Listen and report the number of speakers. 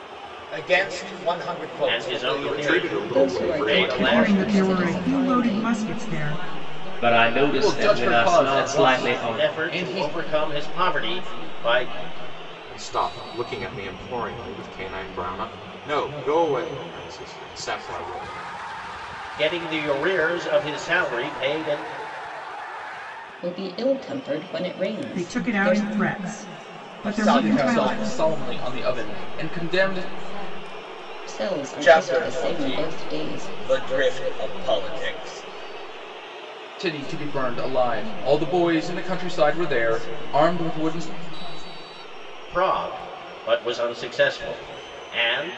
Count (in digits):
8